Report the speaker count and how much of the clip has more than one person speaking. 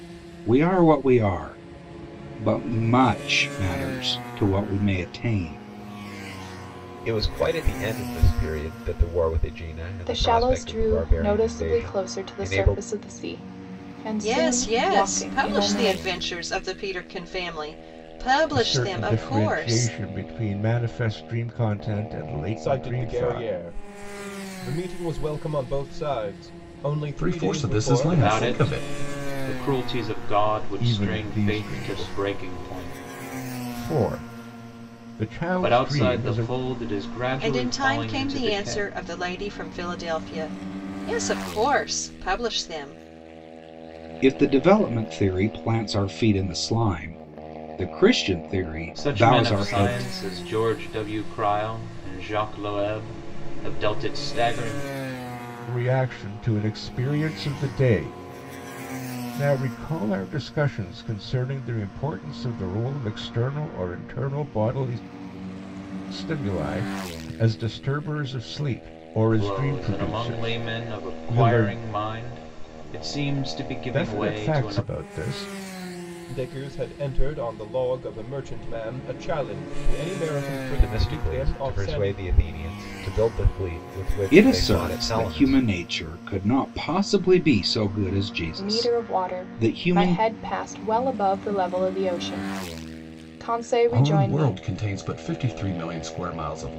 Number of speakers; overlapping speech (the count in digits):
8, about 25%